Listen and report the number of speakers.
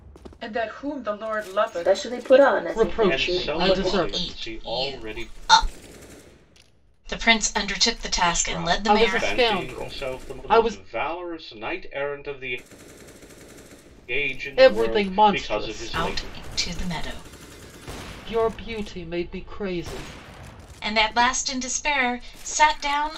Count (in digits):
5